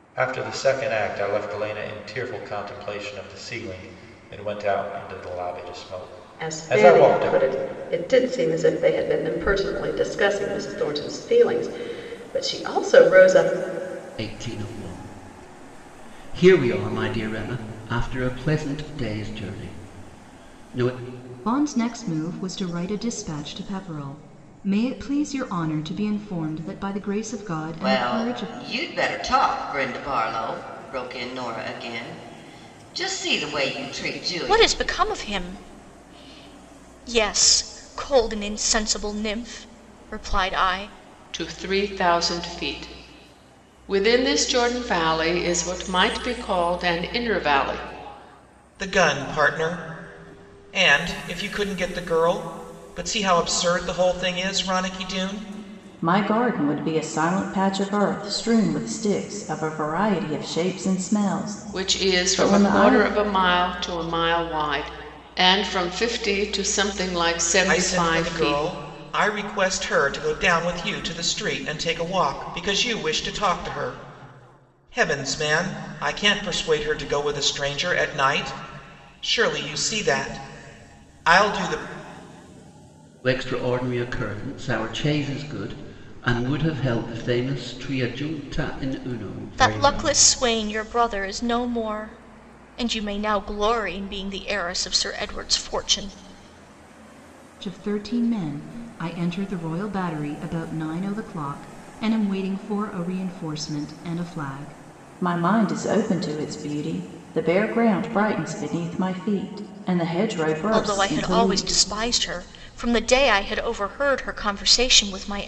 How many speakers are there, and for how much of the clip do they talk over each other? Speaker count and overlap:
9, about 6%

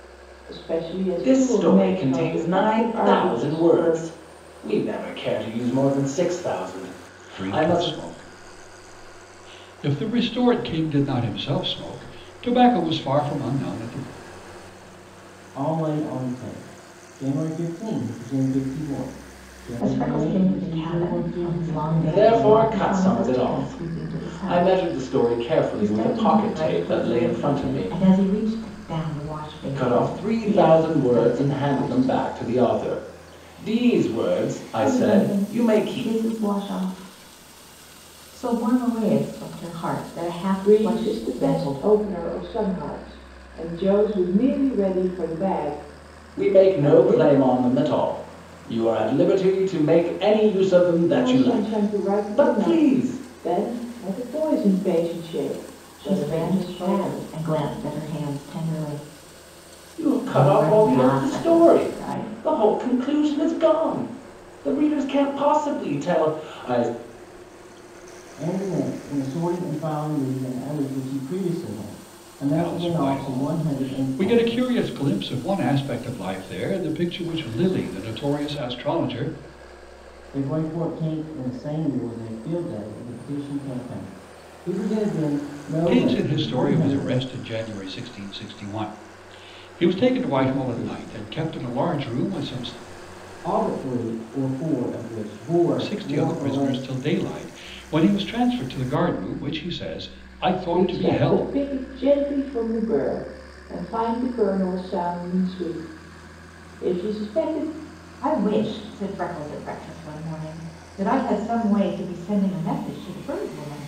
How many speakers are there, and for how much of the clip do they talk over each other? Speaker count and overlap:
5, about 27%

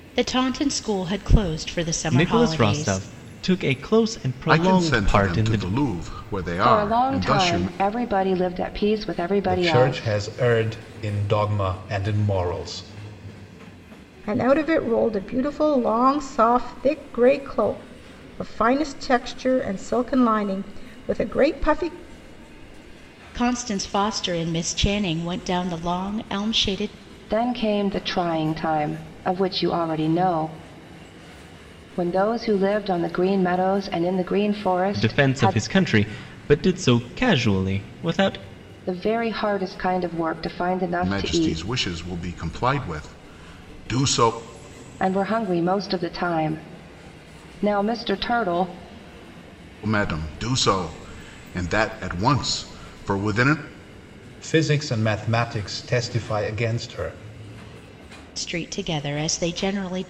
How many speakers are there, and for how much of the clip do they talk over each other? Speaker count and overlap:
6, about 9%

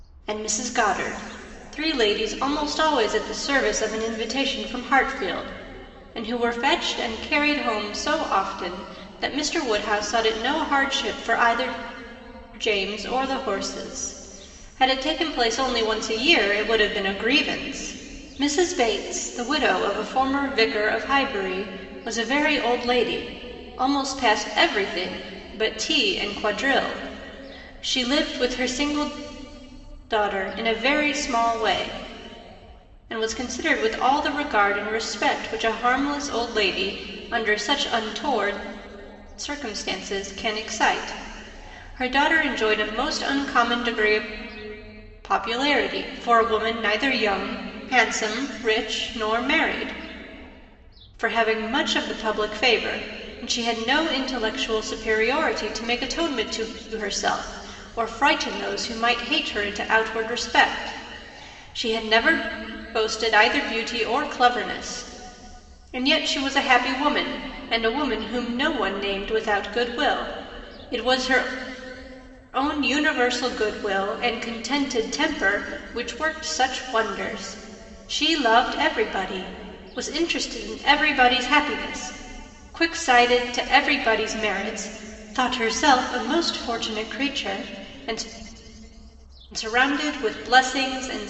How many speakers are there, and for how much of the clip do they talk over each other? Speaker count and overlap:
1, no overlap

